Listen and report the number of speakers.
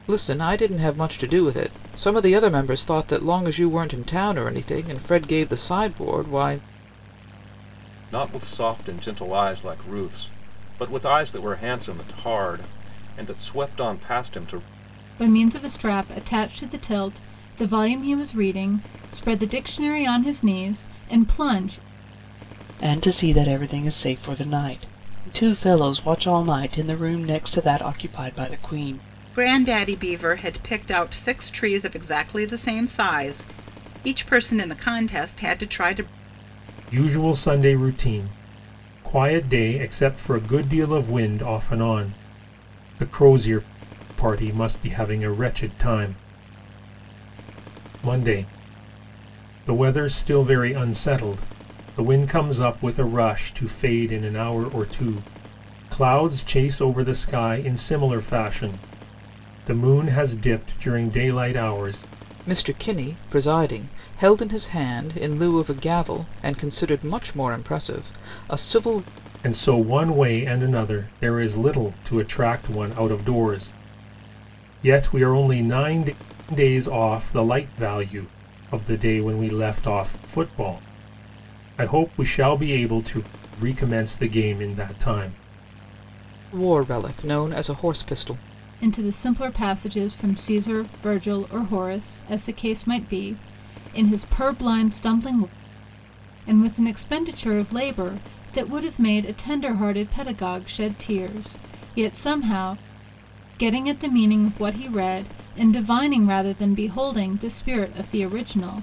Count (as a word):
six